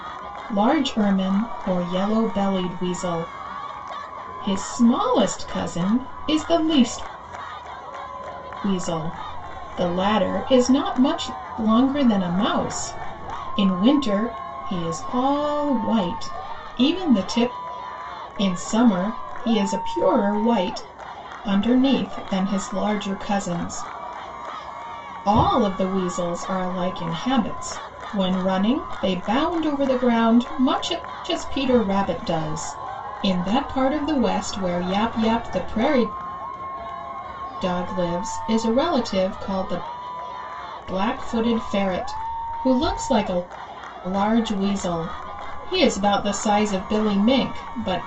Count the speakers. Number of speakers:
one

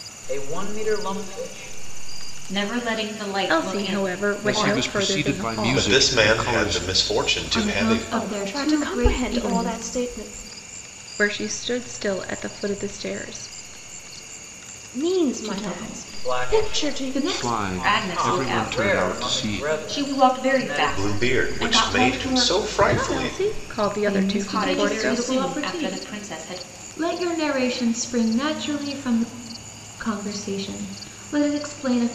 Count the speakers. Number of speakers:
seven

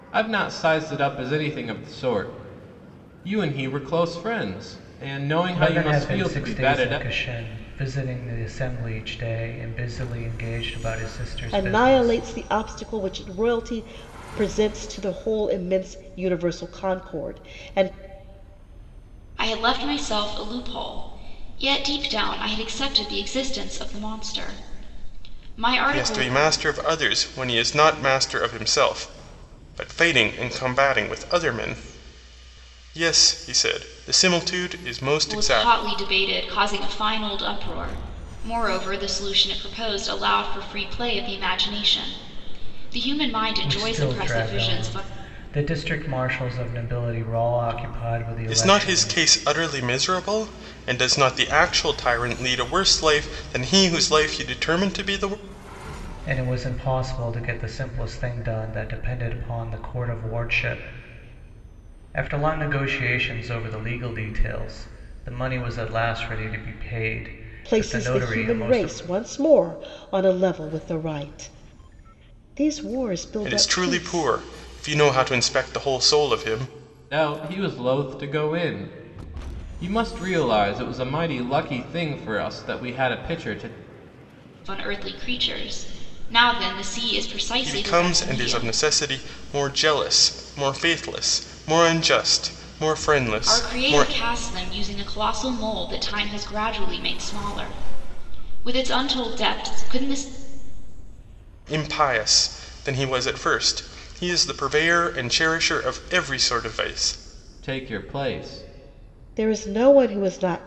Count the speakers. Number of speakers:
five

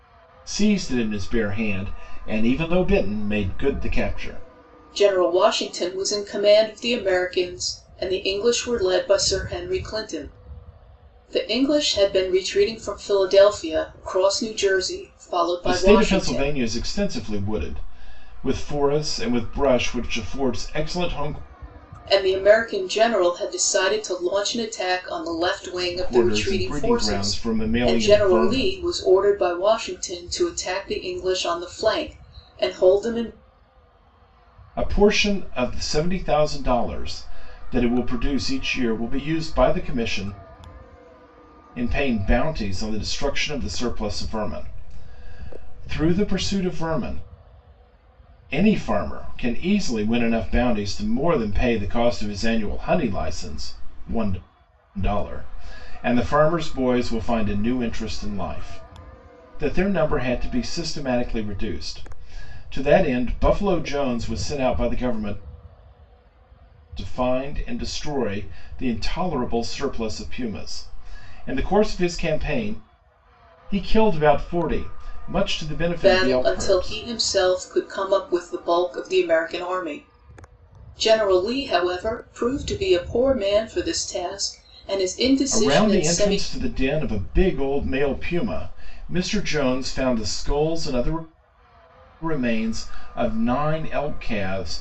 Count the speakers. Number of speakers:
two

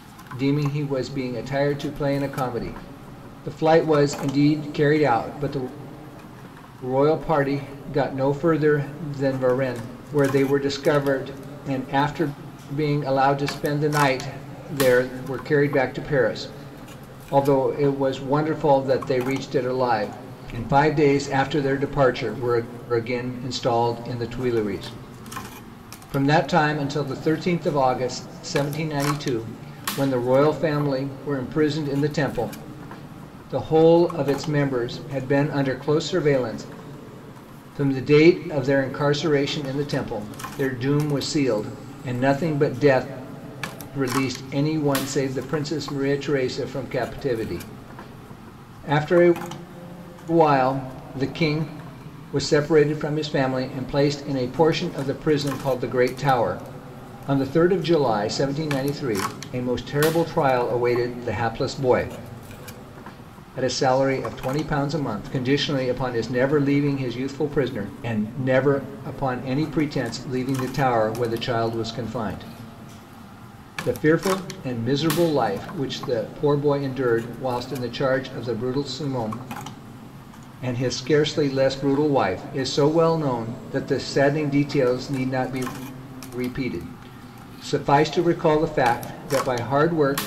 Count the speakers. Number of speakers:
one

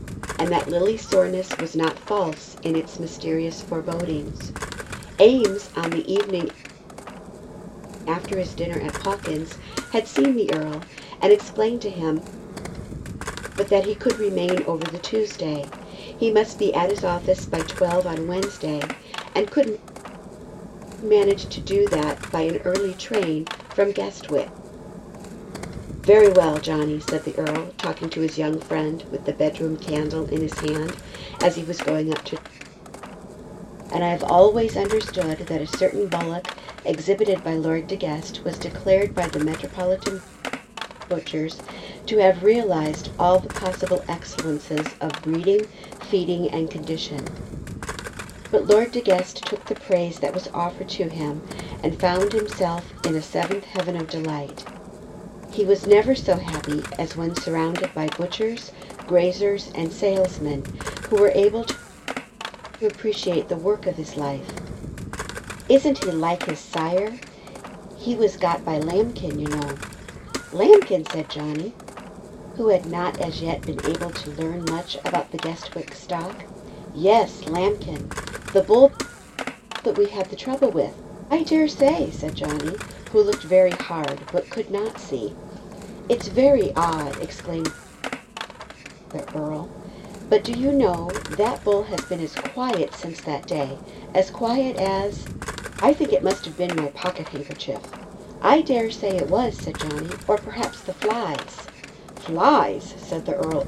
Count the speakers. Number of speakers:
one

